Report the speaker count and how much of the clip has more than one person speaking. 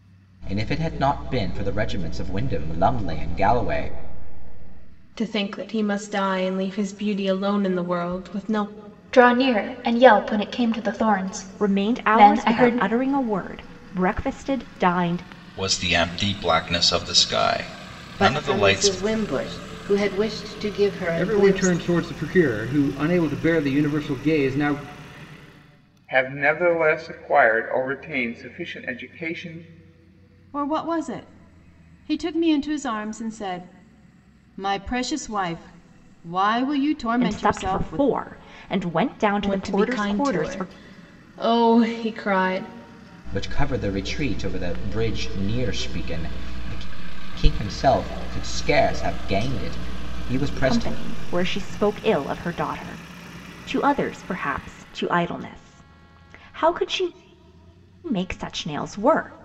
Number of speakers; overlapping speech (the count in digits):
9, about 9%